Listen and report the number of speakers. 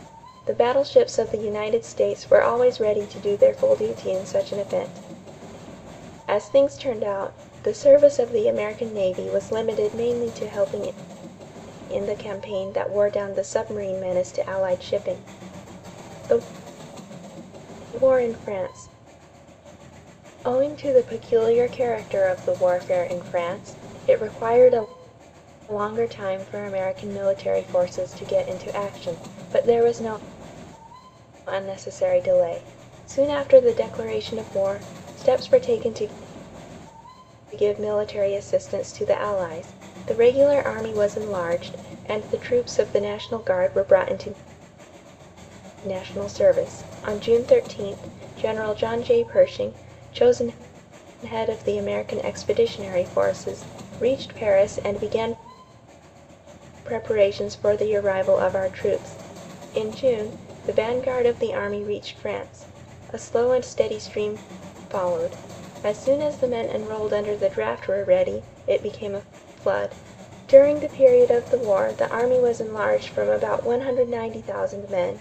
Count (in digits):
1